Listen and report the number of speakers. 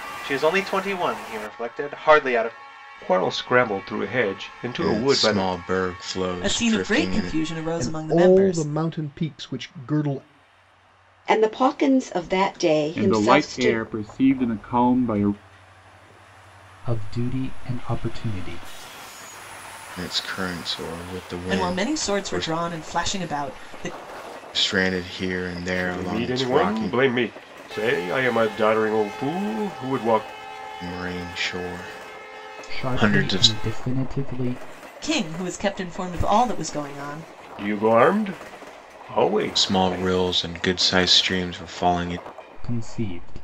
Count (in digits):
8